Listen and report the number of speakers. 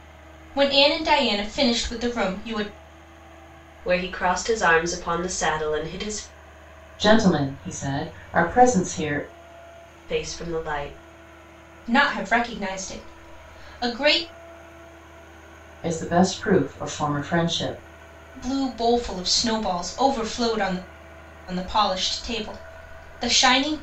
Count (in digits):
3